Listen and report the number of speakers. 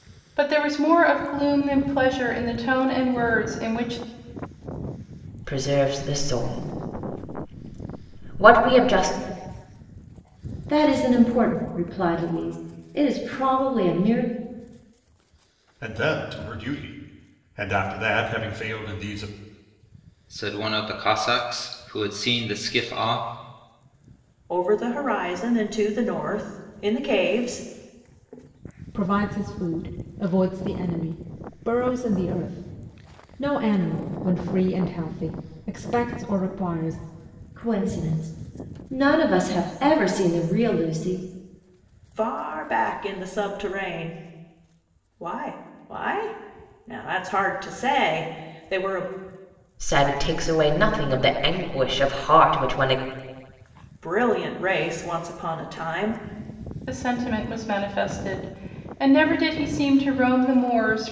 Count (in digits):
7